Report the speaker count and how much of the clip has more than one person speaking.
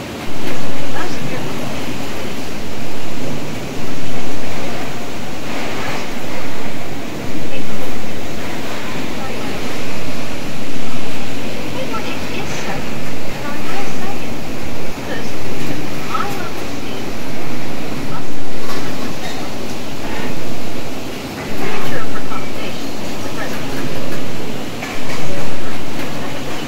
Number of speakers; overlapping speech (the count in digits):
1, no overlap